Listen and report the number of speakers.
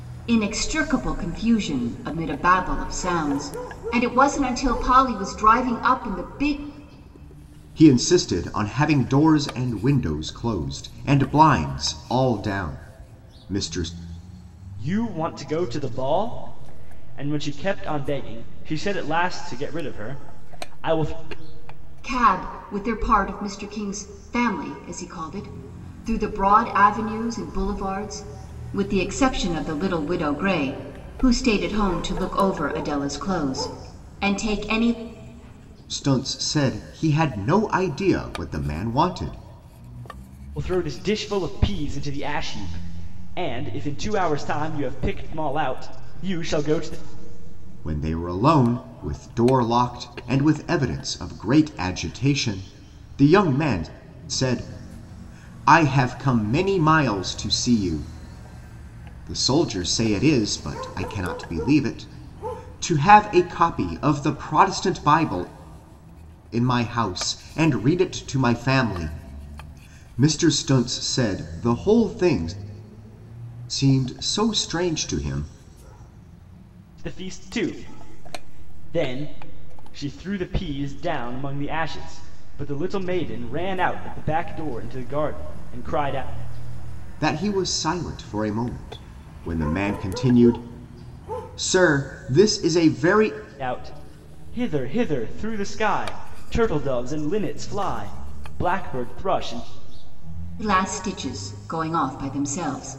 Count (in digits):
3